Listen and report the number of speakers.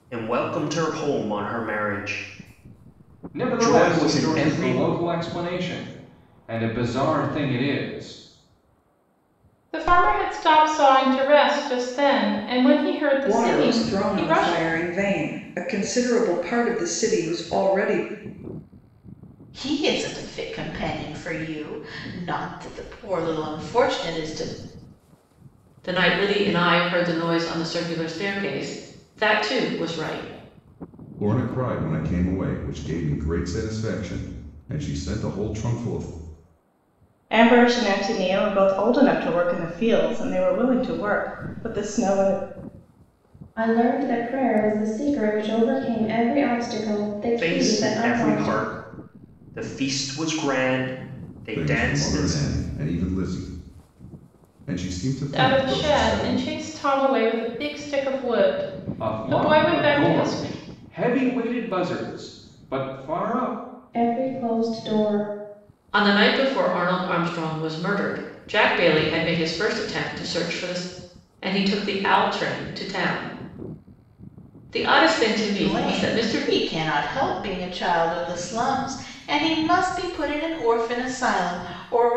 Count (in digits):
9